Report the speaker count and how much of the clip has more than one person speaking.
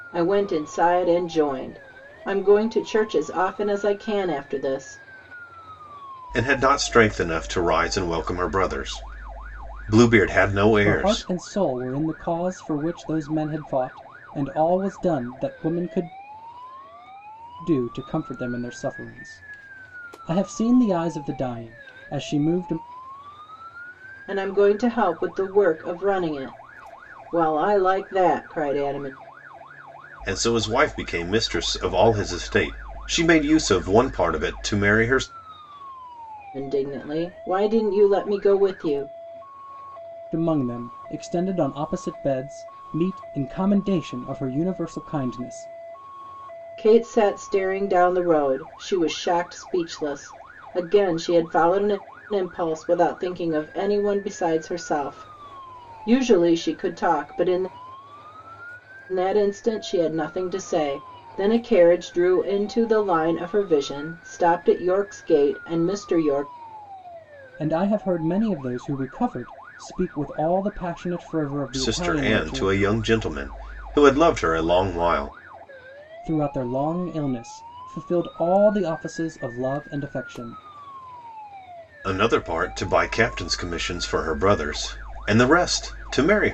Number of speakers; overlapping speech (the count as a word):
three, about 2%